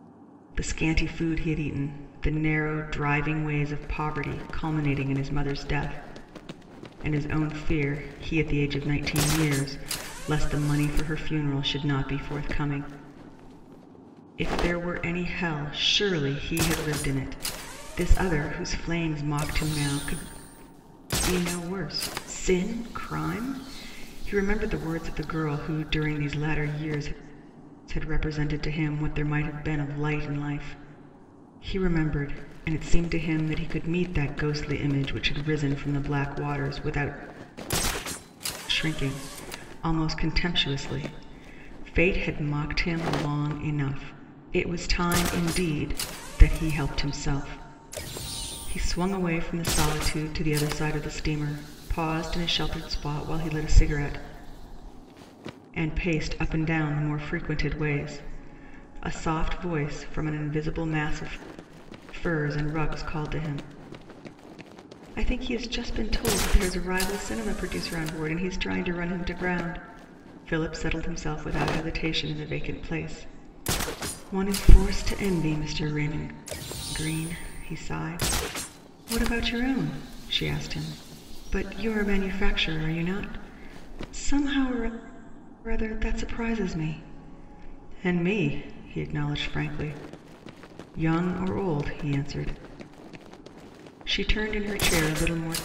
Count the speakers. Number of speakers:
1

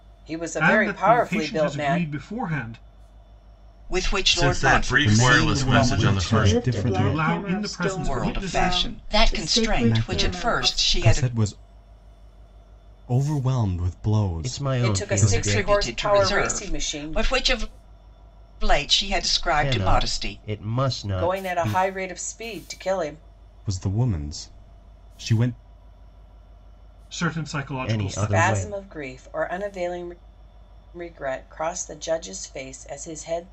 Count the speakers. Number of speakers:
7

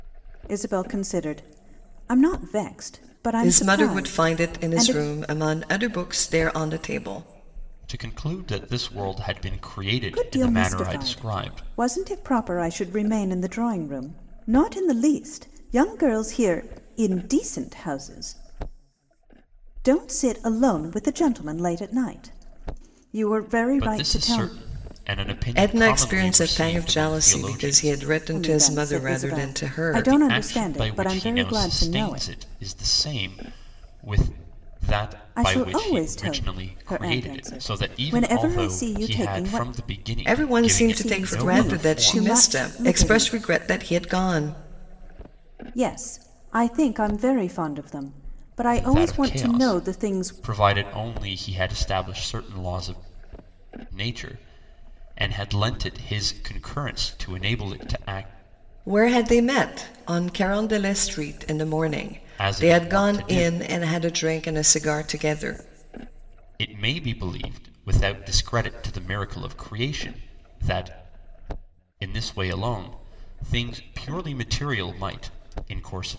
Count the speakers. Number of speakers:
3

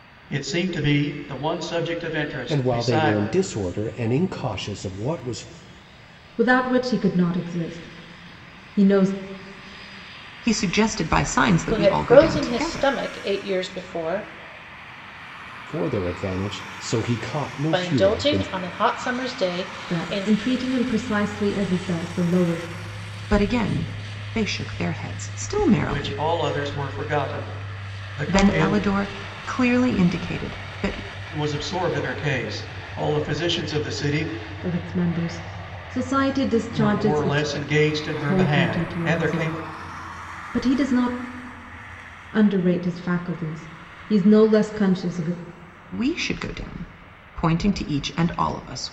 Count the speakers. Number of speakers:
5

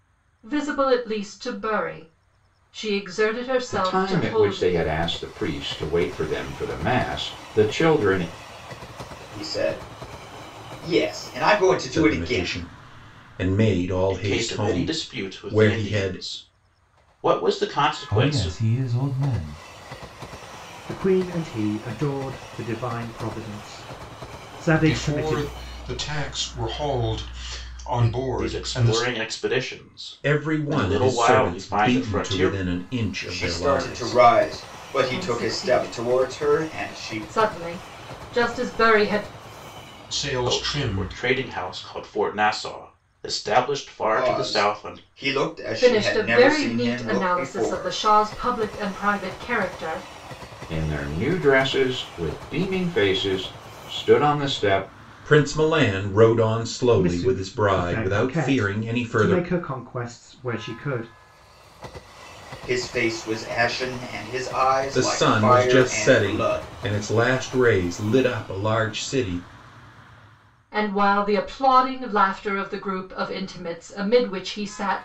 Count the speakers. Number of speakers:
8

